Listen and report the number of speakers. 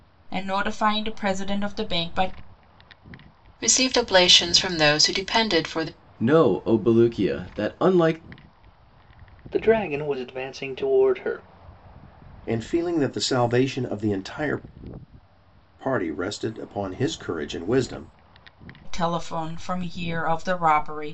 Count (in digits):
5